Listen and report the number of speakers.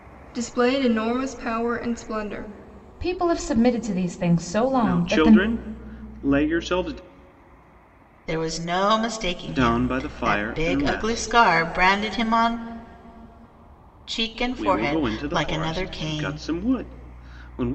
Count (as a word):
four